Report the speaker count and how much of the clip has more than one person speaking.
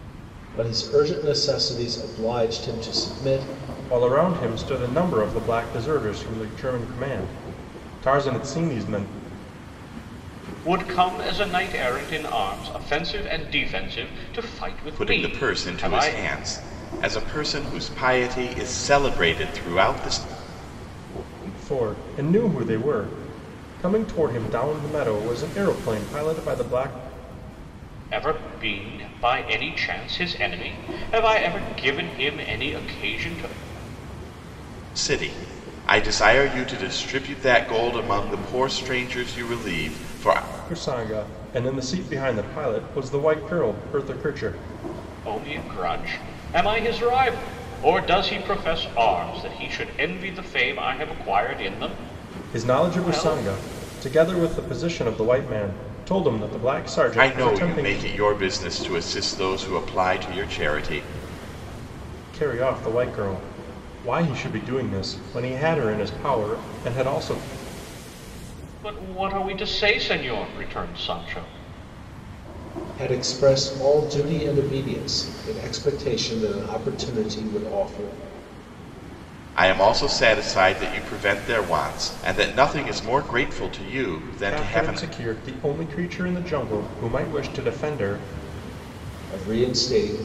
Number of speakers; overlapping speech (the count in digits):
4, about 4%